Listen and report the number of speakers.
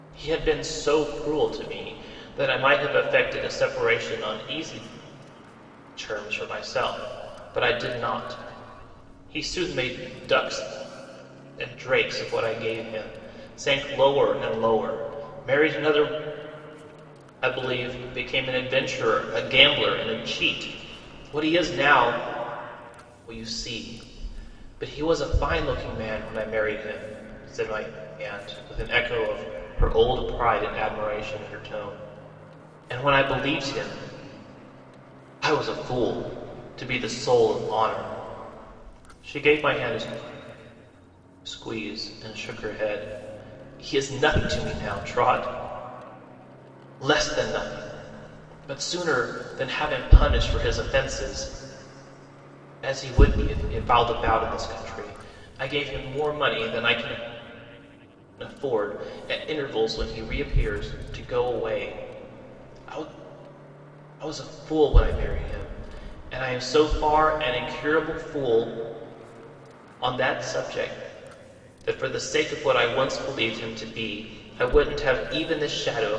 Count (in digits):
1